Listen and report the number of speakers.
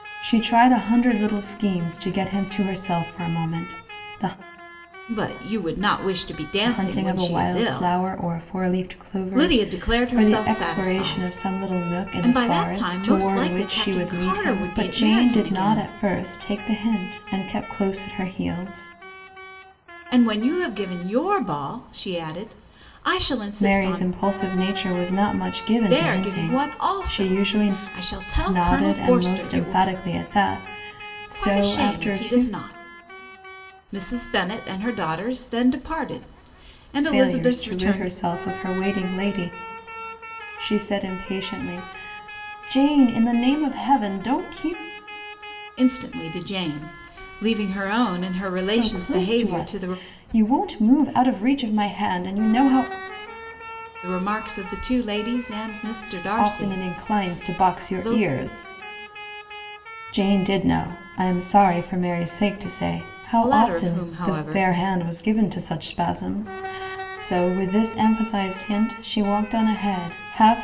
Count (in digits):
2